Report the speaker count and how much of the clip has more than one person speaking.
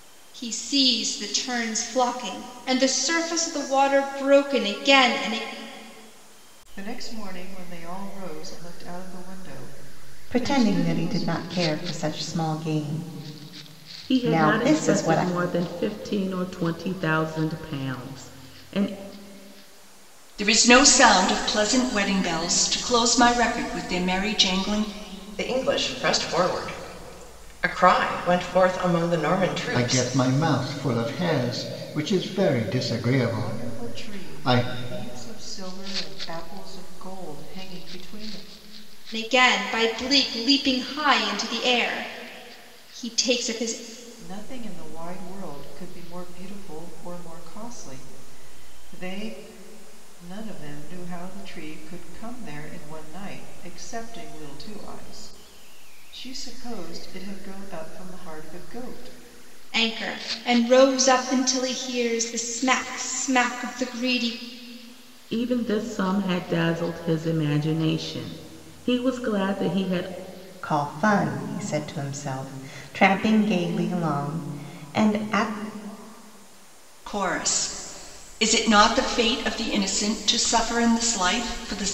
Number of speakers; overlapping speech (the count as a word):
seven, about 5%